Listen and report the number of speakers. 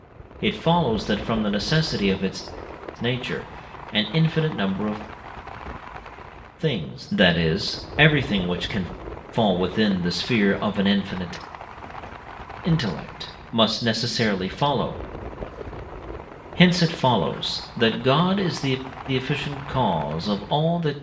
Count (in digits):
1